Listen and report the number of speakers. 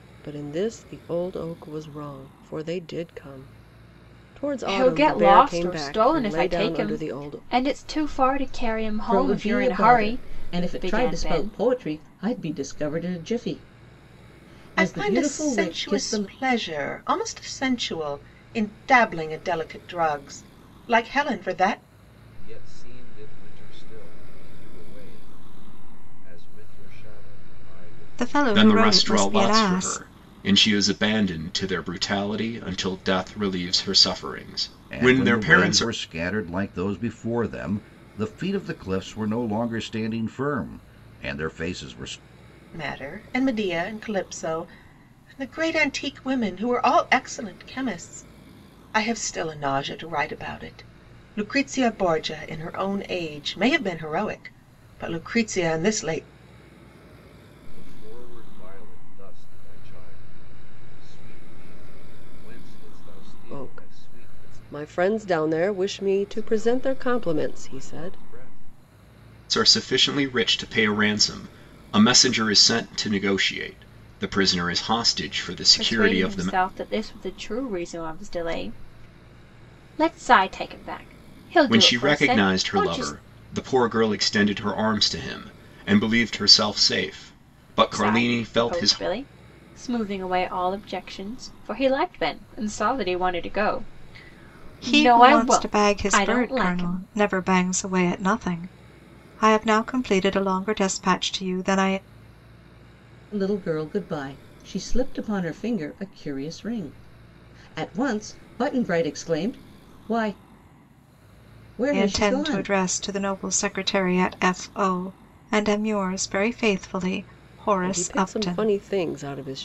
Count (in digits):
8